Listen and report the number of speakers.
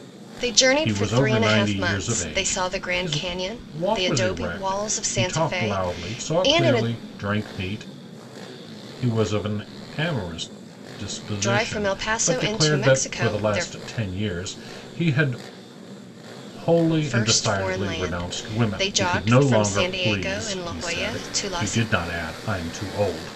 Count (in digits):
2